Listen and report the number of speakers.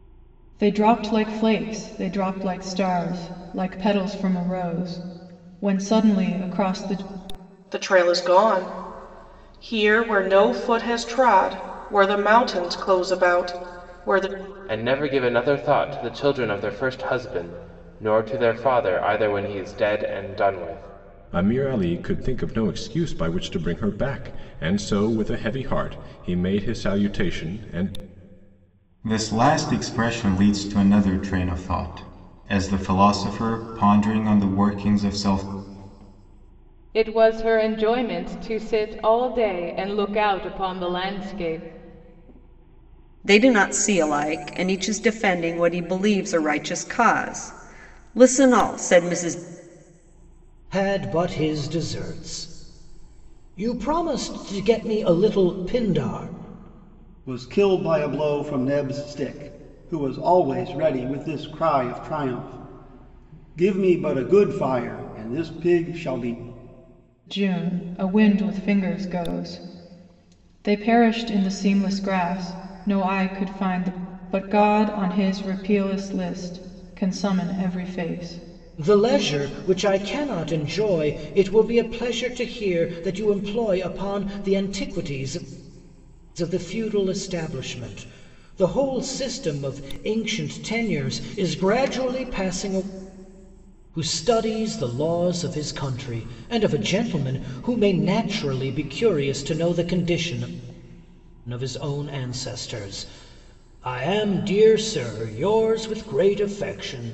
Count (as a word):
nine